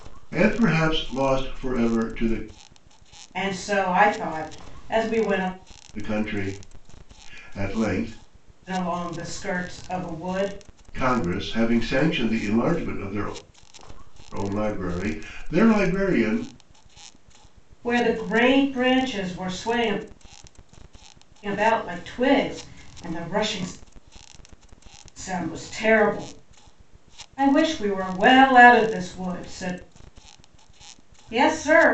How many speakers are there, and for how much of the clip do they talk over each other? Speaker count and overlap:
two, no overlap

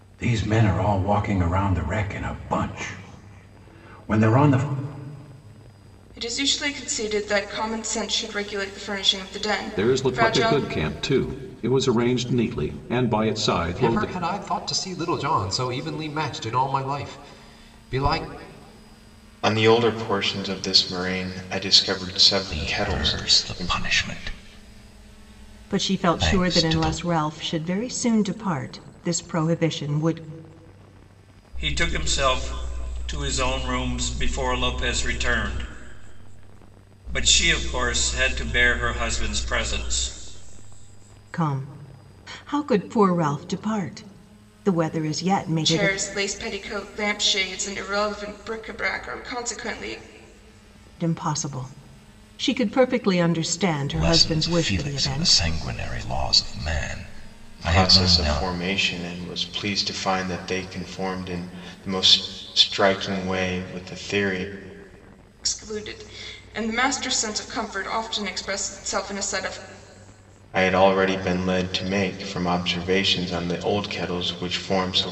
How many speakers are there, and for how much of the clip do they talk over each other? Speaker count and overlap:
eight, about 9%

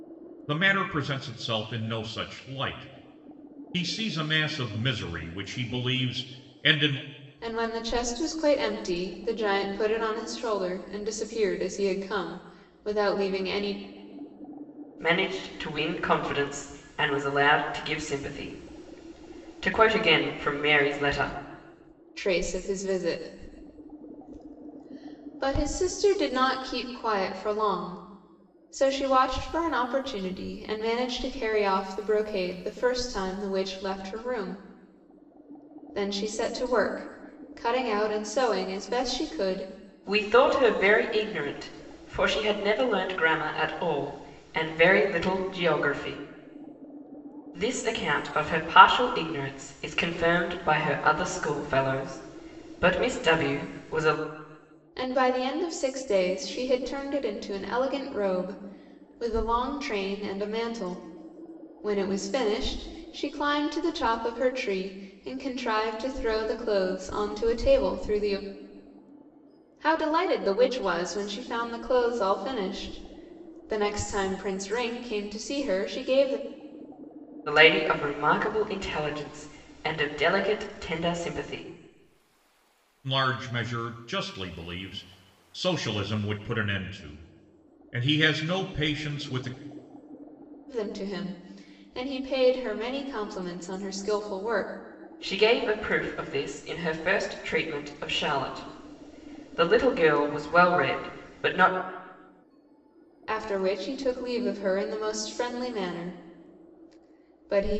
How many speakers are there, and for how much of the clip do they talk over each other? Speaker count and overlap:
three, no overlap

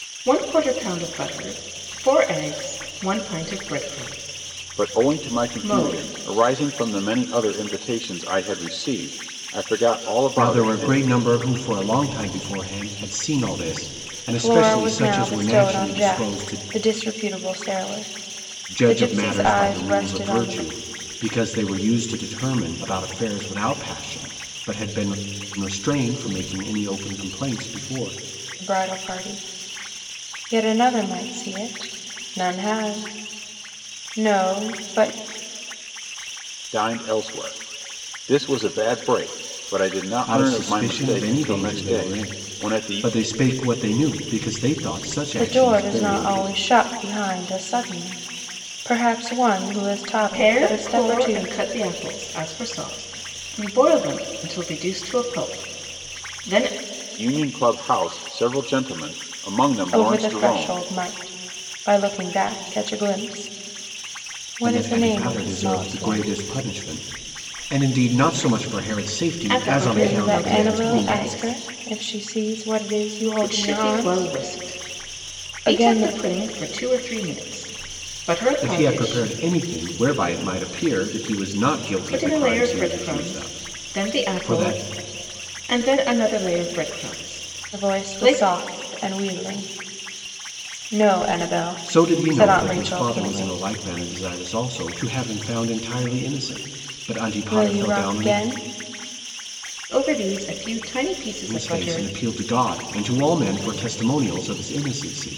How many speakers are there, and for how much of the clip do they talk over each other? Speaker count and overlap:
four, about 26%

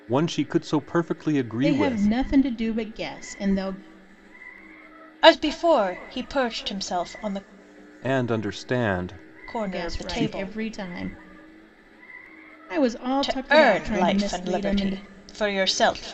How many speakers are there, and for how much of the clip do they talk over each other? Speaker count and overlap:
three, about 22%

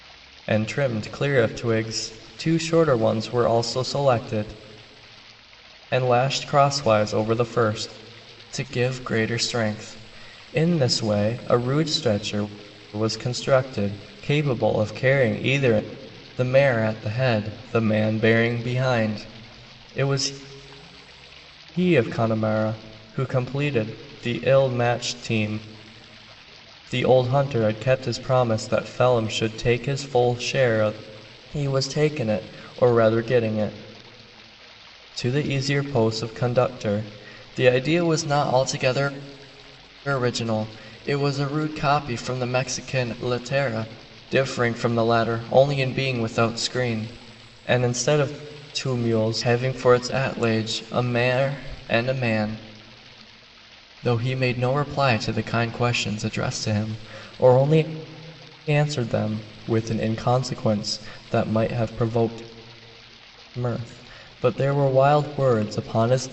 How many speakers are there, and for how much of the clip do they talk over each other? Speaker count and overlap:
one, no overlap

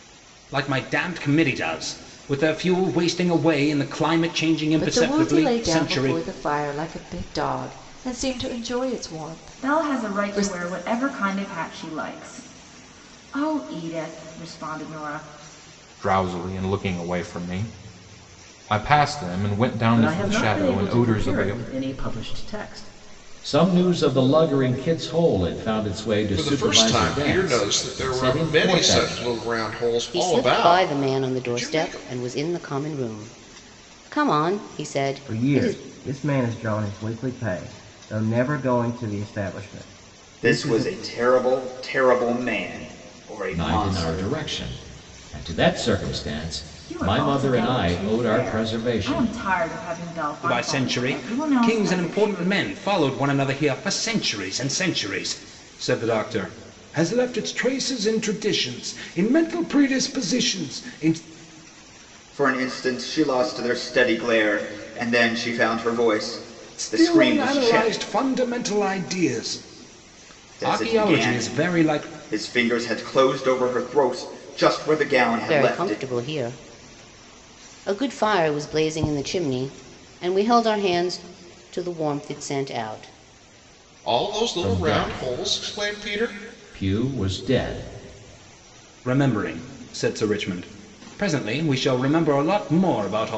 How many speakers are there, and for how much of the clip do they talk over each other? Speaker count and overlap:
ten, about 23%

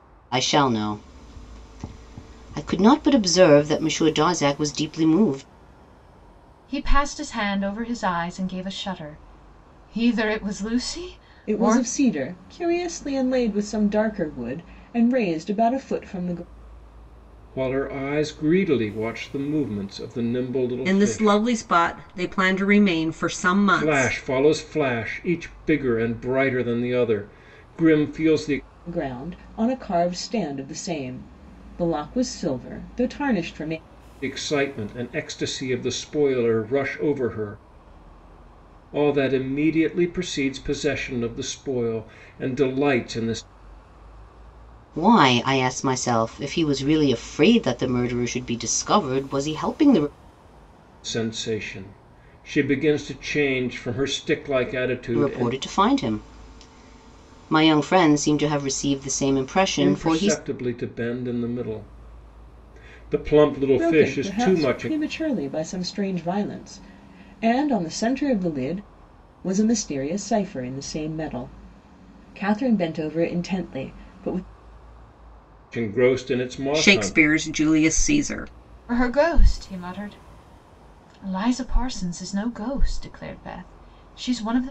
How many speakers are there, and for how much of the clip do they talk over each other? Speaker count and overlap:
five, about 5%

